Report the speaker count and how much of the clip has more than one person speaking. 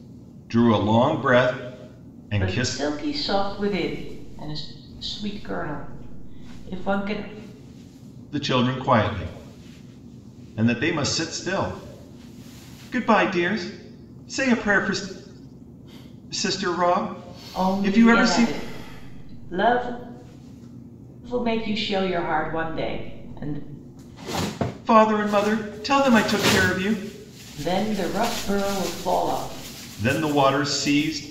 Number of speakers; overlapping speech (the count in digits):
2, about 5%